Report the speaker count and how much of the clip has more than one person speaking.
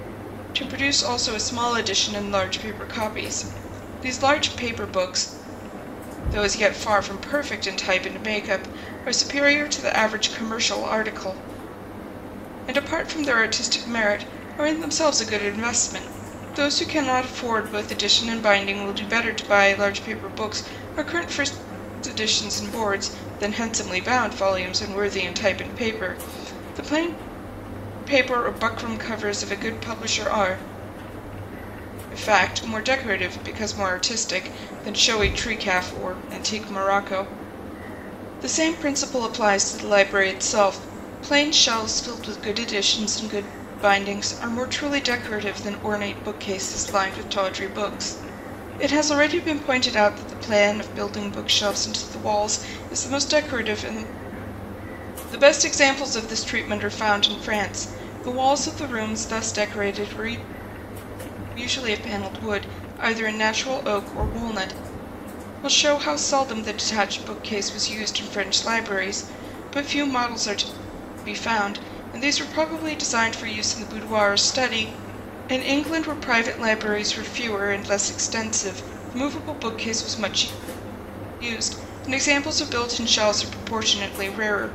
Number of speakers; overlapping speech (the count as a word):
one, no overlap